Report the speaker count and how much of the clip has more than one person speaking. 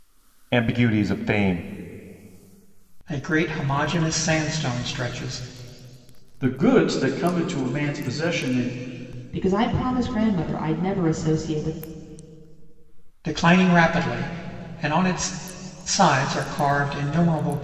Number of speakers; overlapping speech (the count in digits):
4, no overlap